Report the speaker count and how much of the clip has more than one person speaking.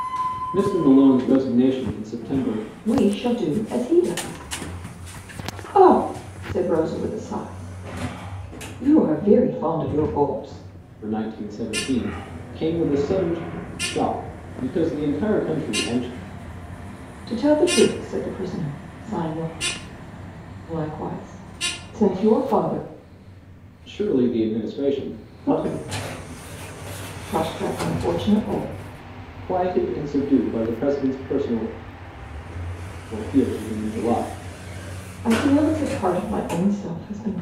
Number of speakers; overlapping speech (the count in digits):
2, no overlap